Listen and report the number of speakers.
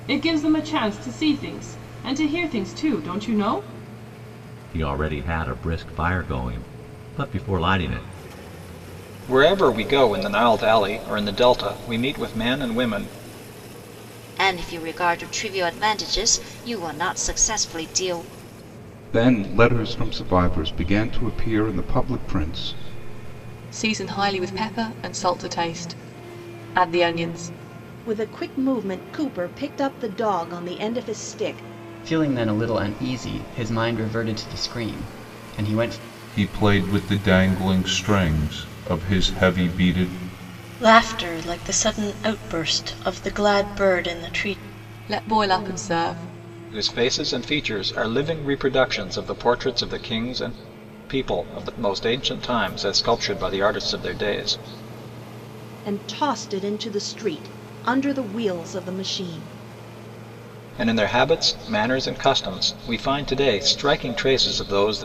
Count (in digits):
10